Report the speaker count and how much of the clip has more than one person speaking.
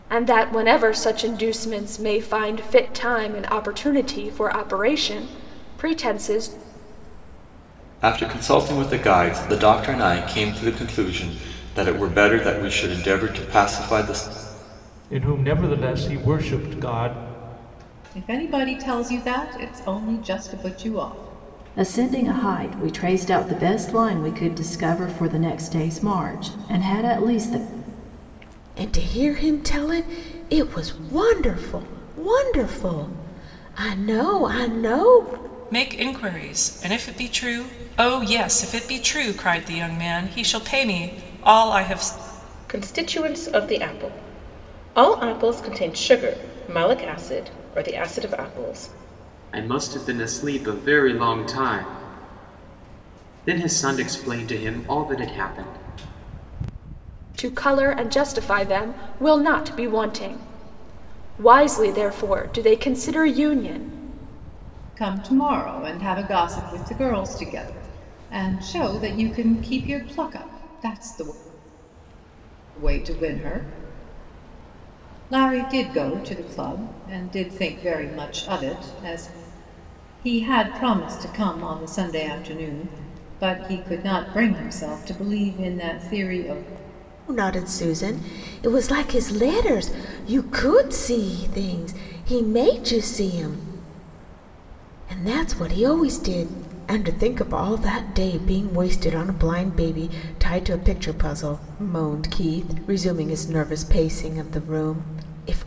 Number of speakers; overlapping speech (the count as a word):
nine, no overlap